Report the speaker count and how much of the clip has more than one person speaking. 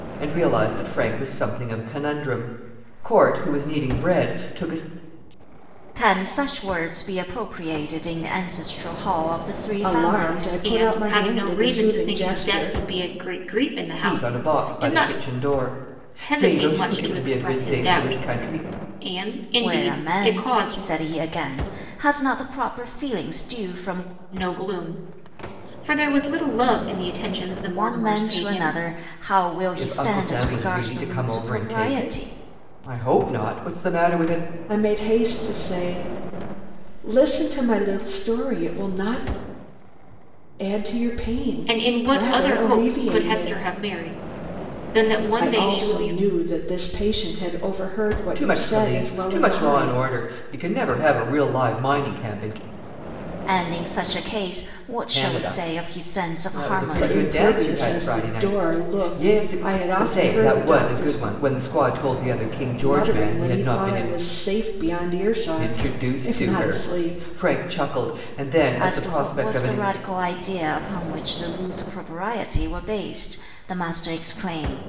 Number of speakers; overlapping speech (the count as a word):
four, about 35%